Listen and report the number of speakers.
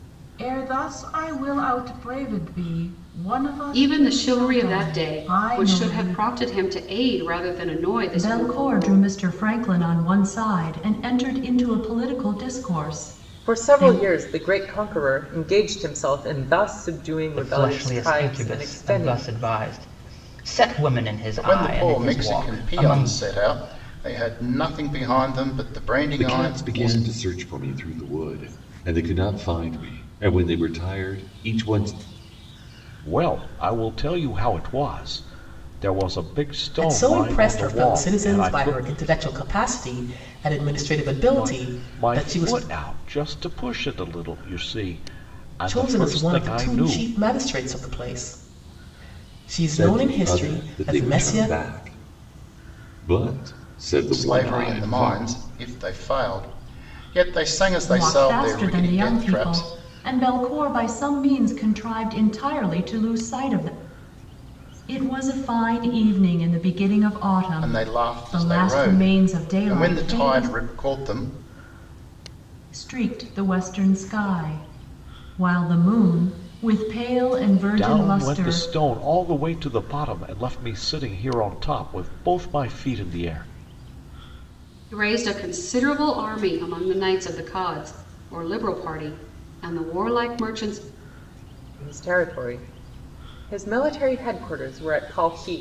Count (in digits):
9